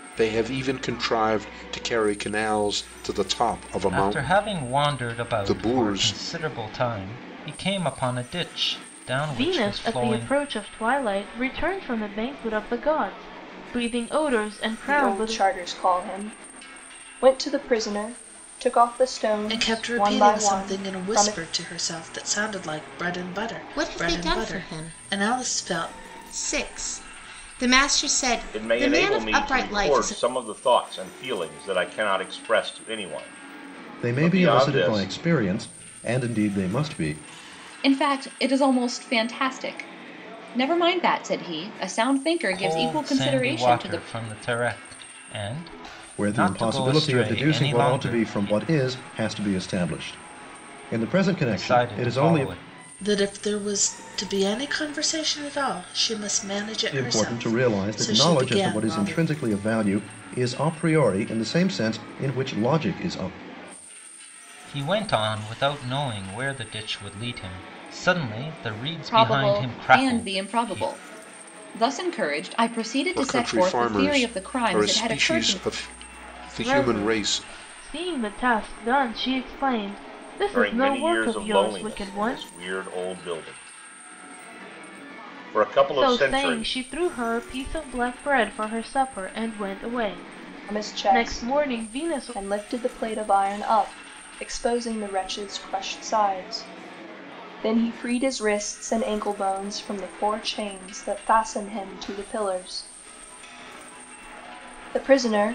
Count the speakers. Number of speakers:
9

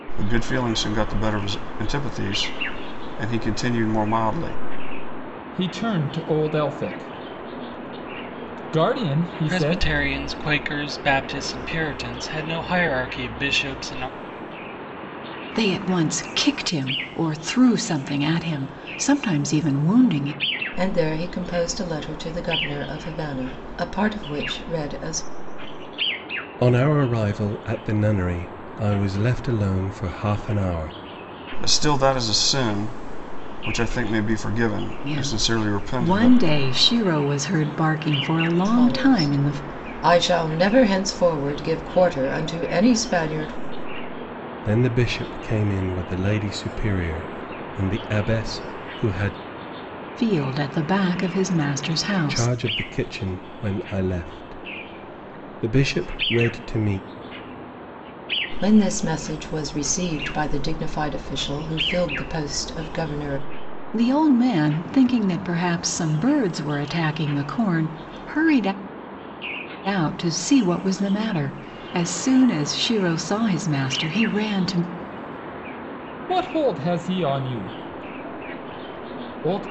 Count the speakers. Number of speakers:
6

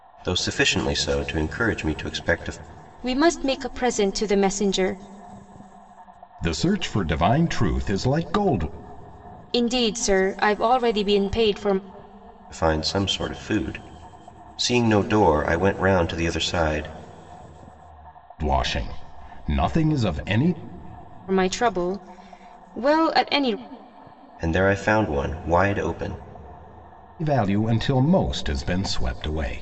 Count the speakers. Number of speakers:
3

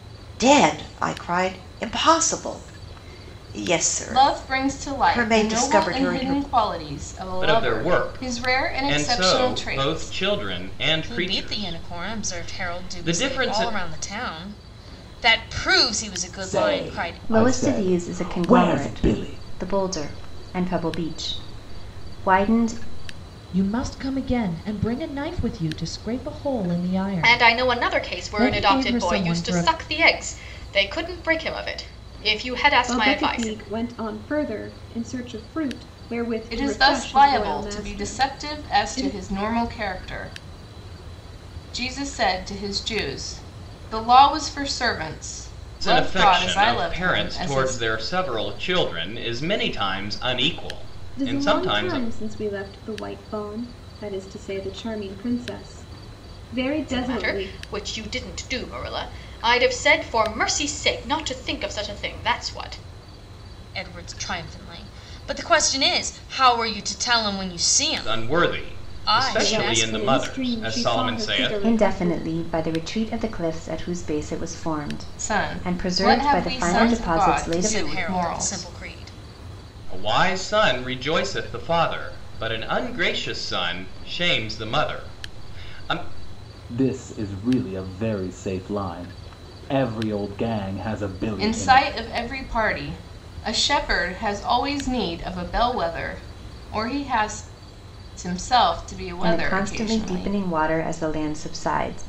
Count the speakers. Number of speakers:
9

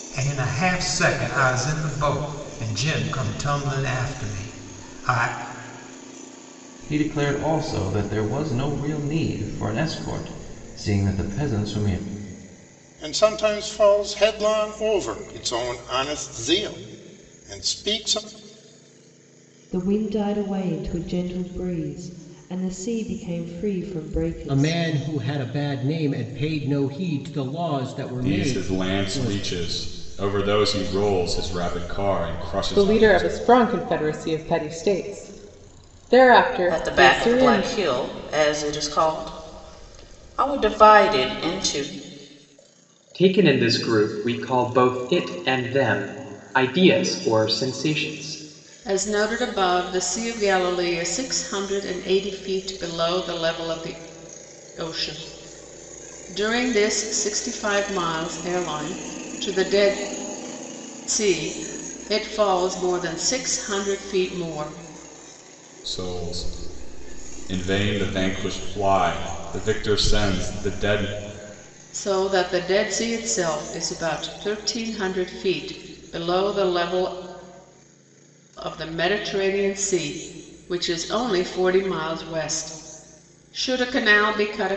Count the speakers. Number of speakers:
10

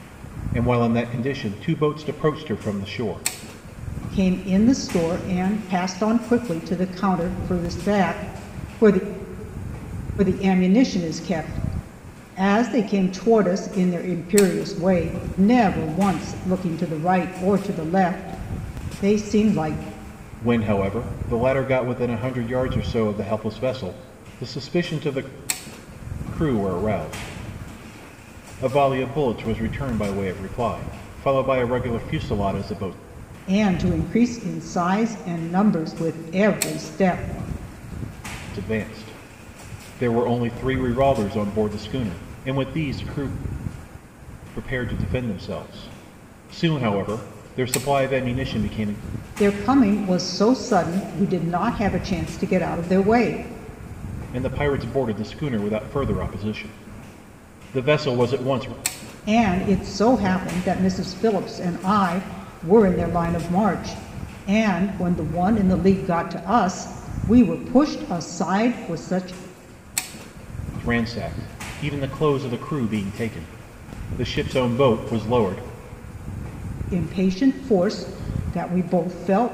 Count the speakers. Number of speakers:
2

